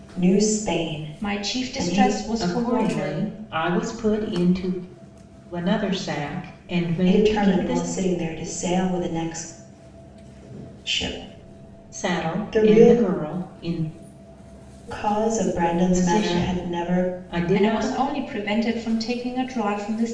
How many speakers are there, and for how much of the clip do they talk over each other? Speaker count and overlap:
3, about 26%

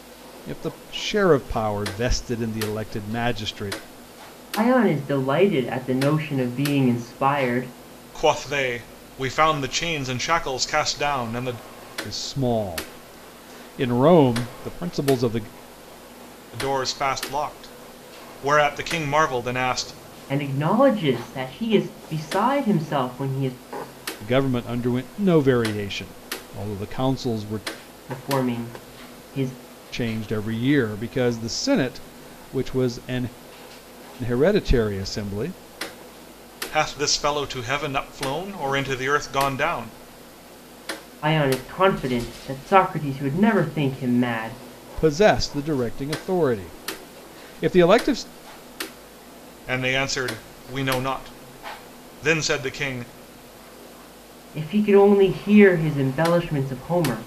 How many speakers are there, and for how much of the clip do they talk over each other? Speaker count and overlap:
3, no overlap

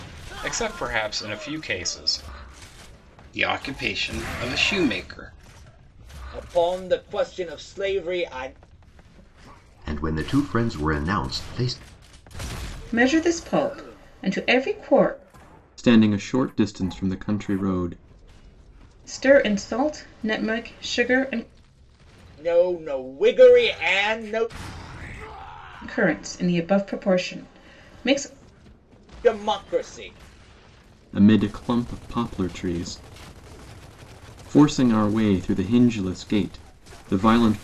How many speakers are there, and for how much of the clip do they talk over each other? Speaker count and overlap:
6, no overlap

